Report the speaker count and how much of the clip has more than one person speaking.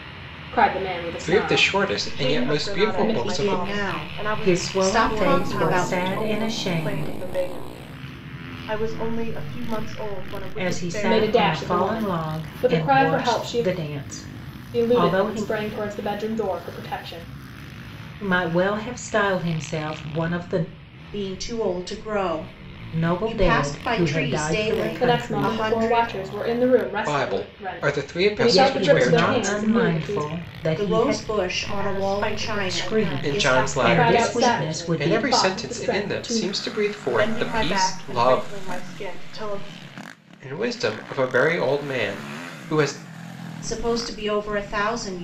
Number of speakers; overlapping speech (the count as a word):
five, about 52%